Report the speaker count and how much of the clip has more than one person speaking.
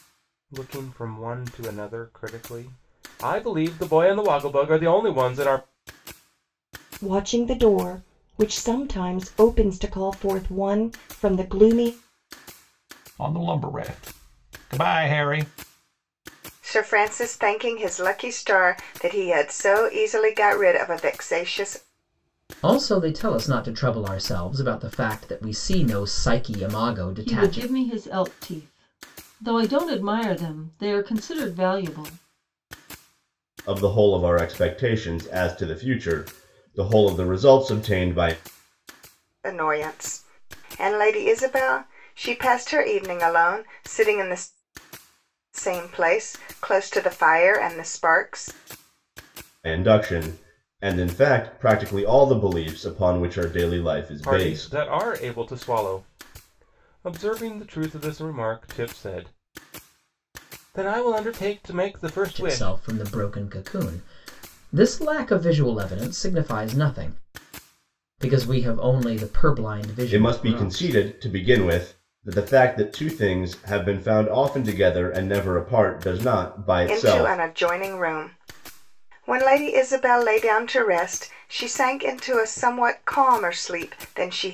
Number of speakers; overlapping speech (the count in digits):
7, about 4%